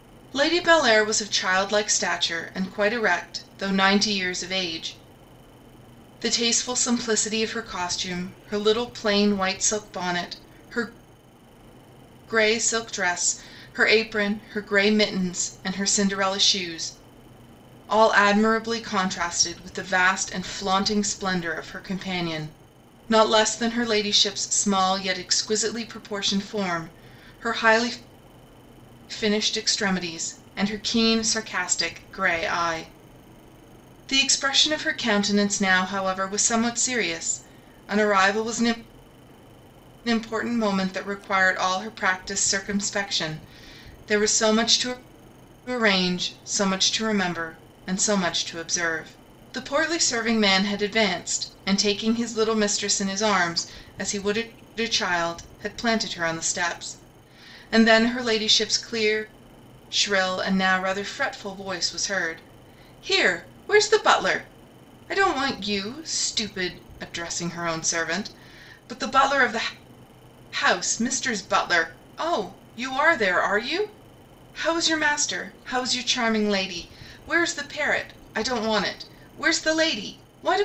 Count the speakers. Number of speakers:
1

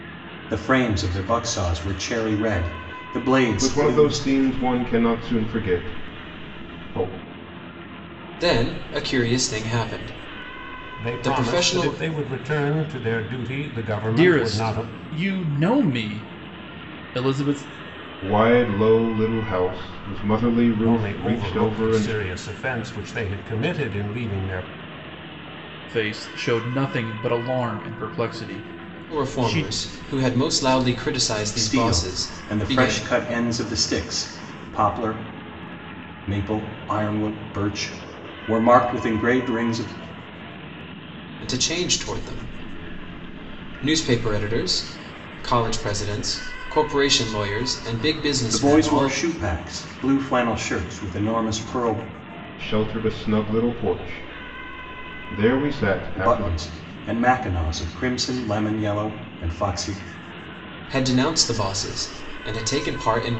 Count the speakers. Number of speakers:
5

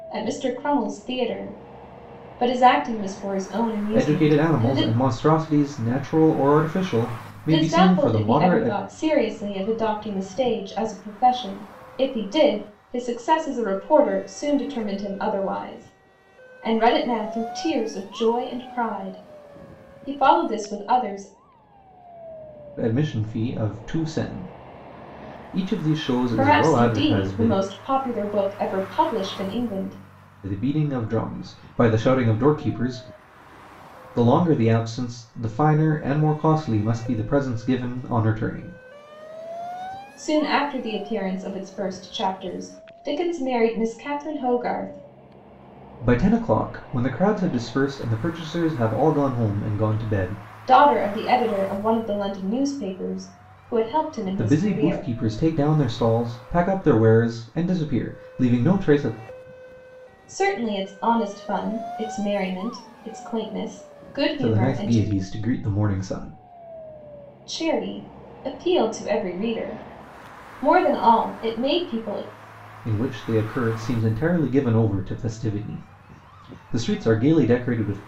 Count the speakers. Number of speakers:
2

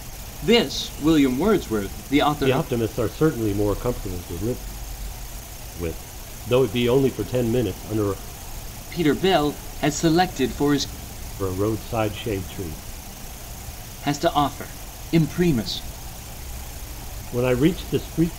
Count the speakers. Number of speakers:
2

